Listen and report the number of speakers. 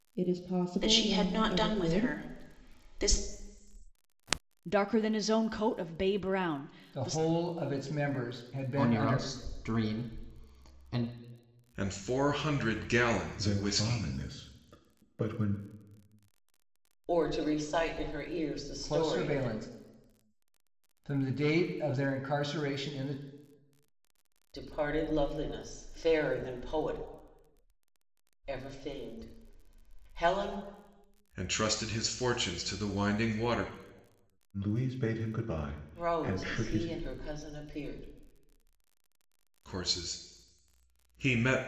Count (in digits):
8